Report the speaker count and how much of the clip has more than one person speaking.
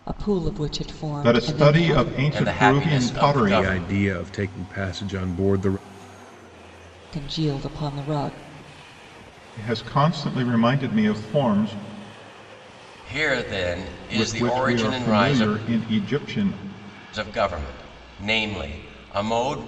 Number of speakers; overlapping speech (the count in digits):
4, about 21%